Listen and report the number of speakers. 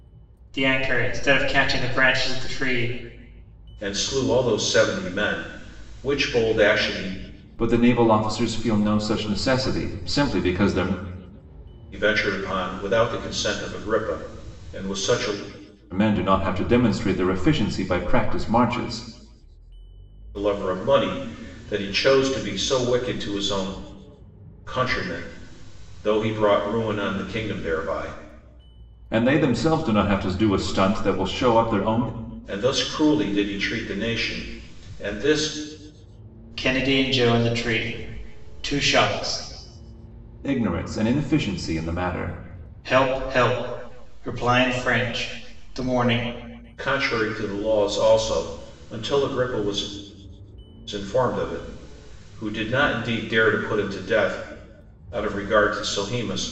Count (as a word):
three